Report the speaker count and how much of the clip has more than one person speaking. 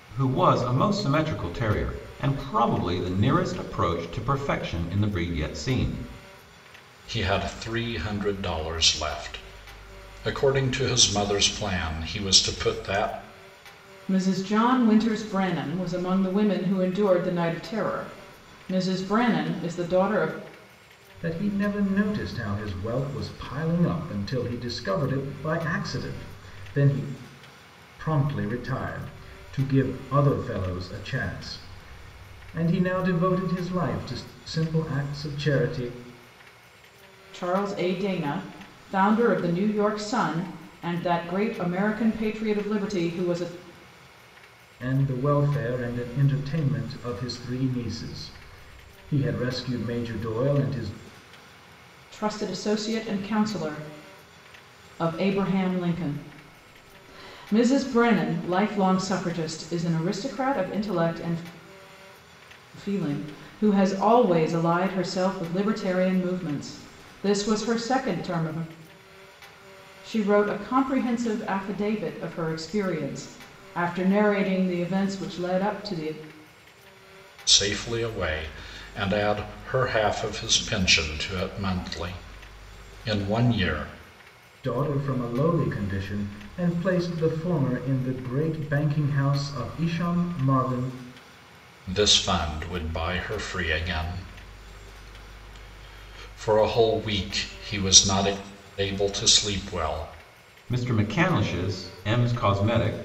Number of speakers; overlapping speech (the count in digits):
4, no overlap